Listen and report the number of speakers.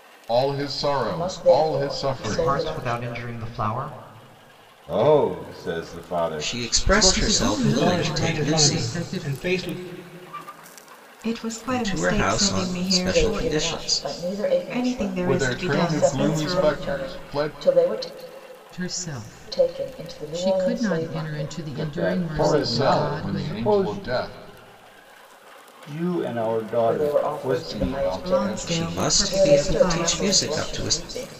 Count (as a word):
eight